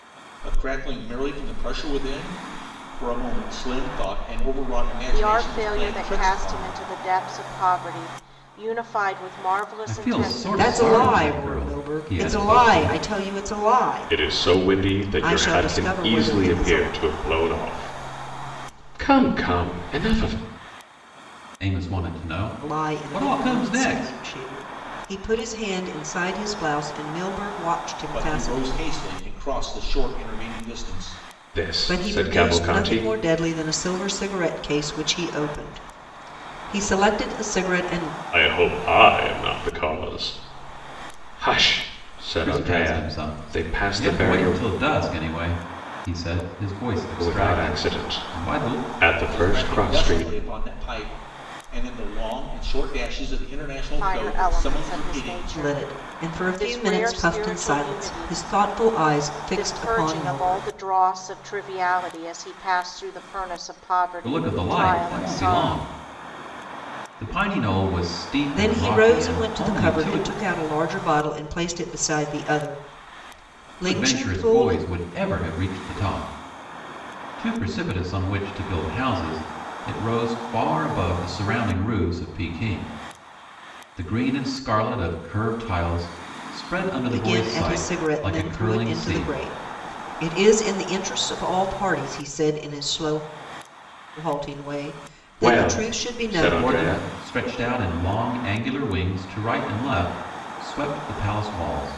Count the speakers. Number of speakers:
5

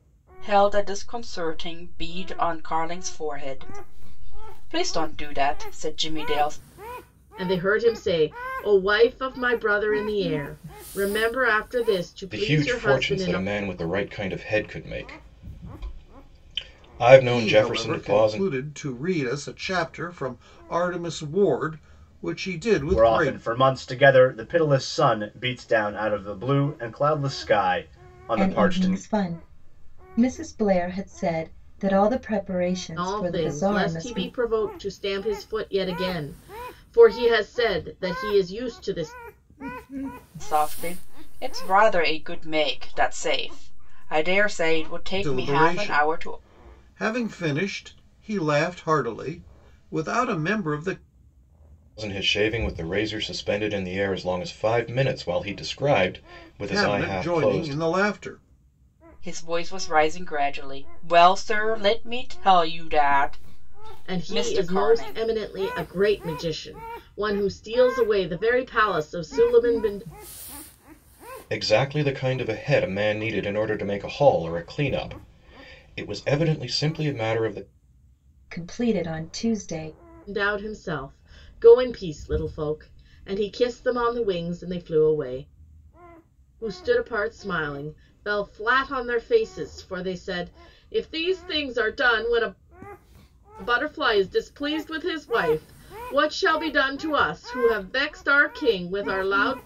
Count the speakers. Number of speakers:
6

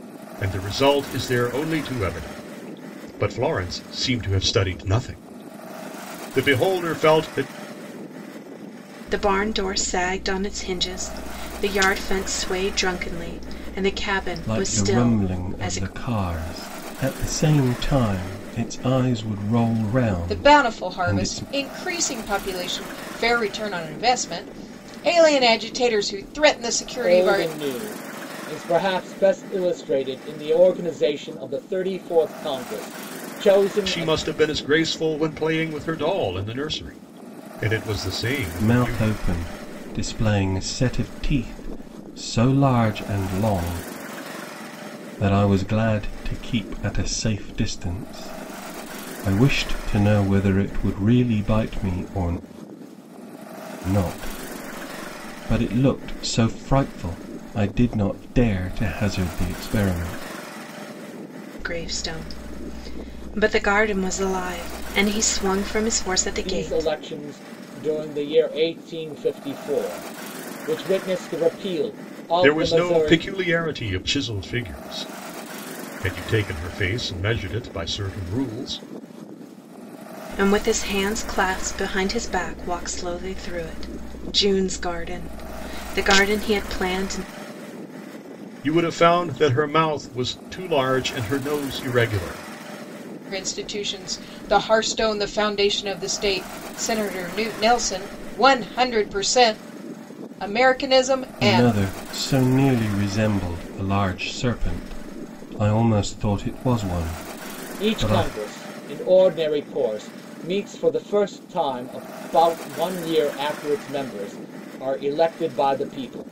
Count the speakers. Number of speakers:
5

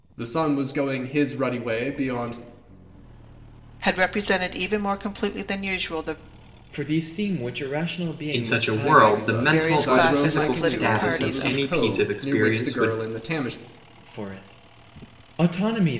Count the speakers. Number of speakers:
4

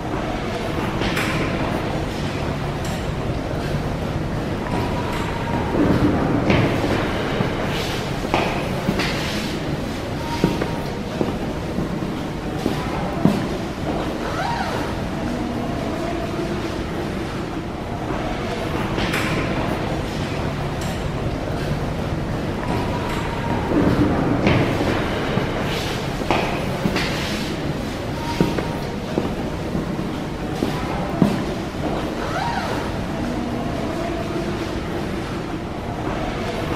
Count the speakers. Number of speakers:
0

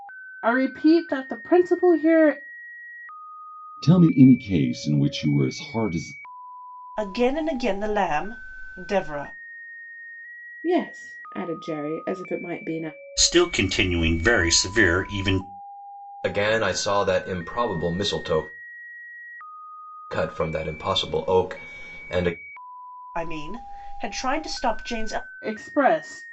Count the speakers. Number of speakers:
6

